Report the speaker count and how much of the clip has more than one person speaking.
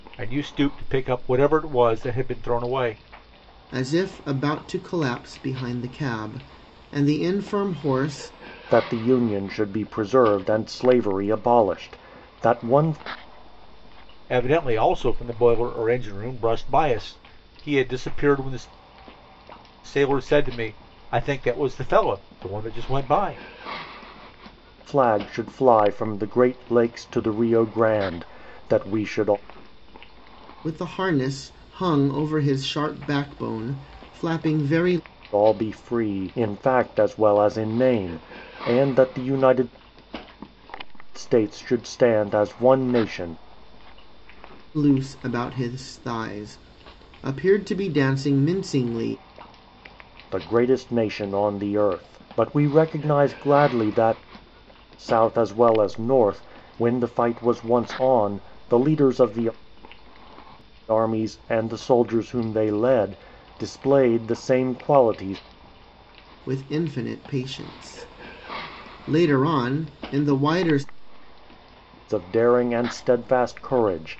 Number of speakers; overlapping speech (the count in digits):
3, no overlap